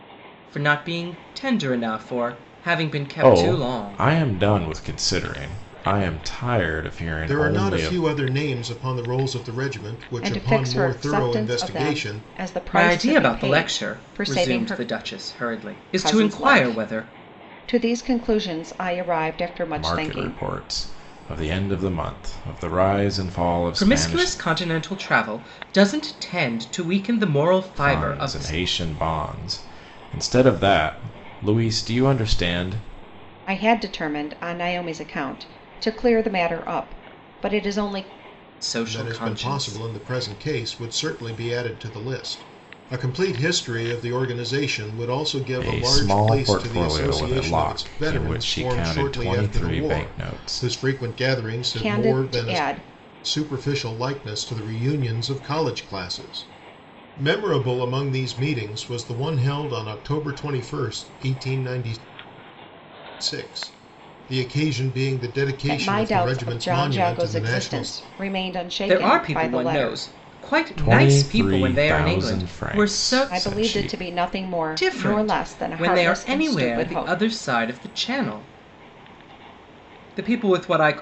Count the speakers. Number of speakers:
4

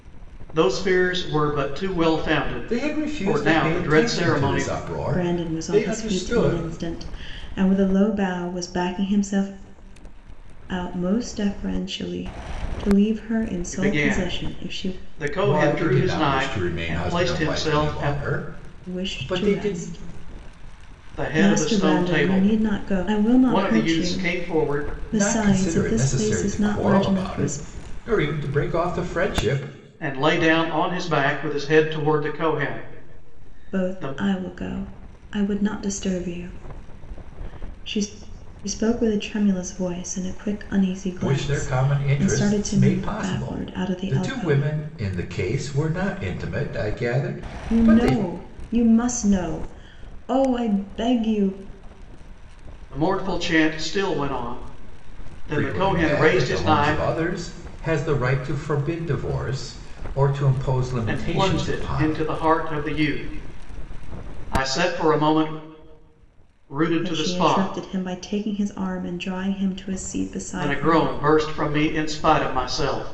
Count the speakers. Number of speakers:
3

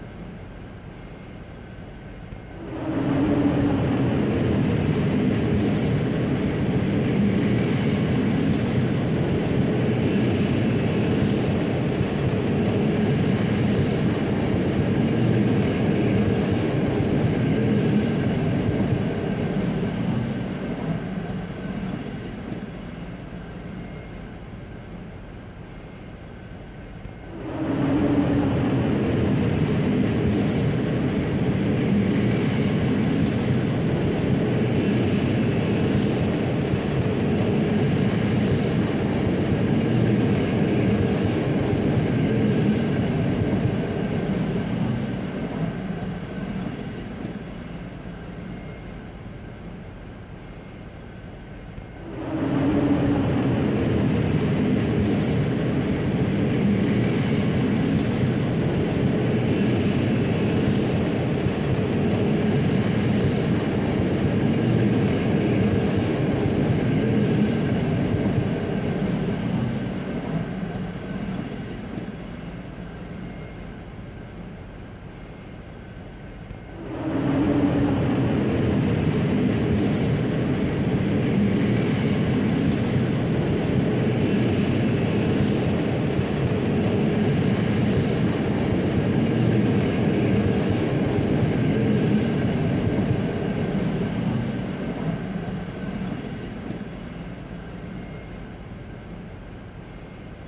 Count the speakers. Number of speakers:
0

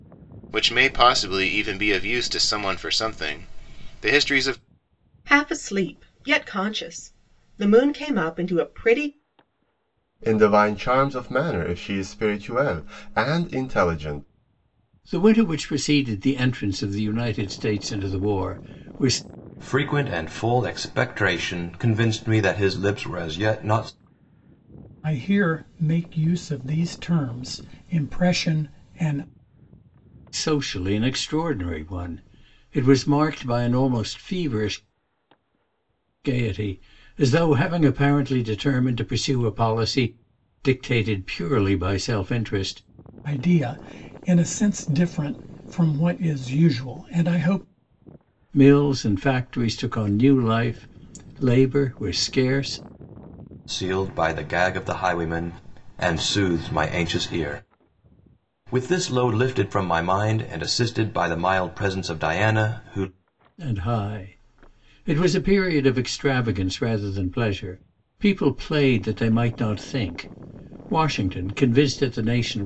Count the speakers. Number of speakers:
6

